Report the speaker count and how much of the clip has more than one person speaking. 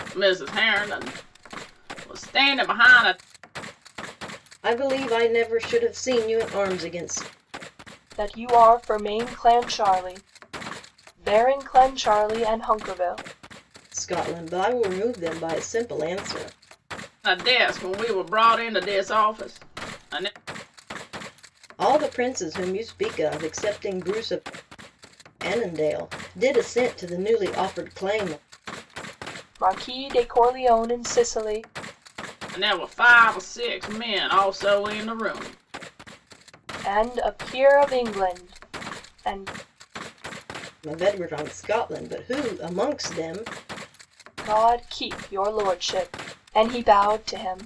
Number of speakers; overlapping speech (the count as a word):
three, no overlap